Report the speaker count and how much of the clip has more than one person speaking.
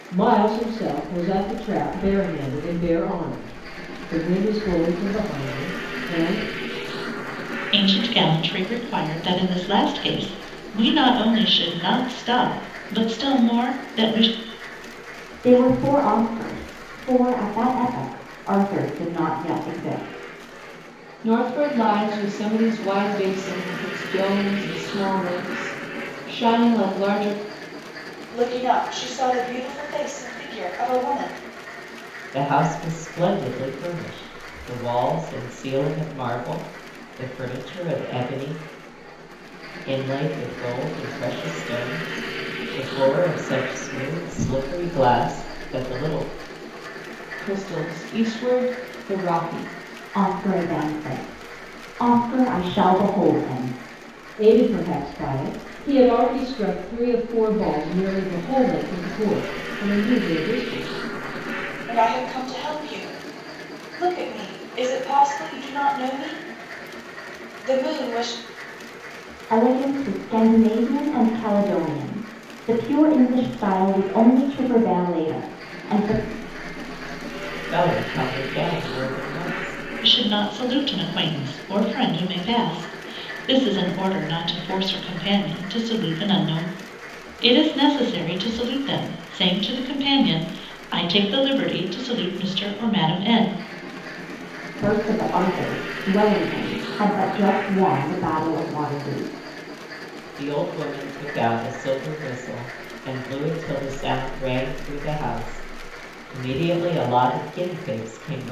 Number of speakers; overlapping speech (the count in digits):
6, no overlap